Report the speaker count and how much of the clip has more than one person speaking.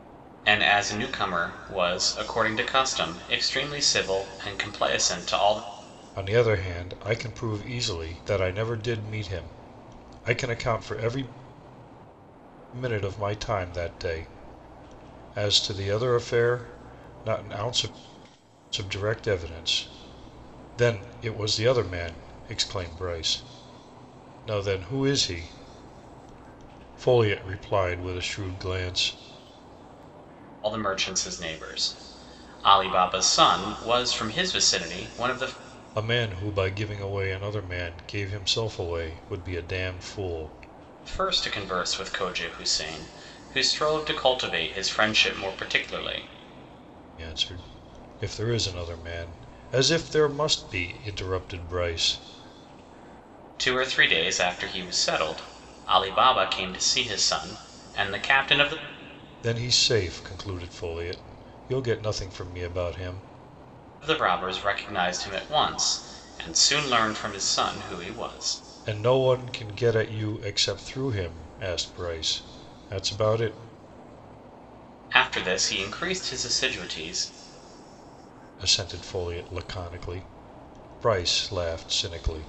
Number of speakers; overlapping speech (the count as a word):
two, no overlap